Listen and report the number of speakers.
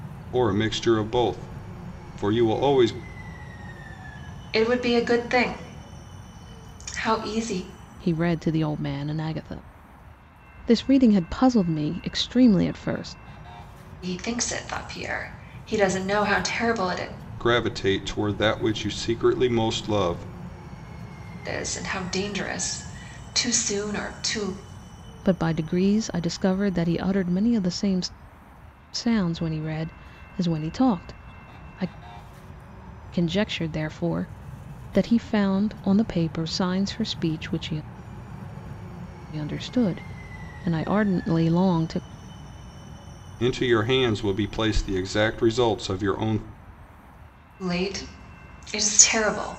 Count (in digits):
3